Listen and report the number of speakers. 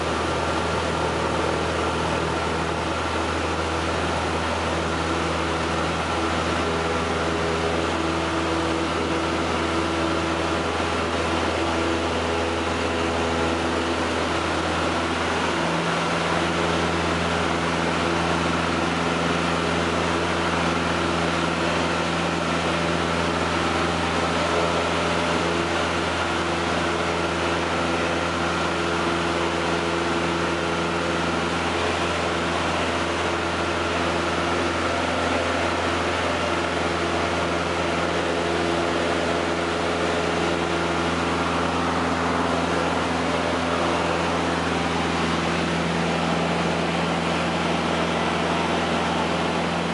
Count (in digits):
0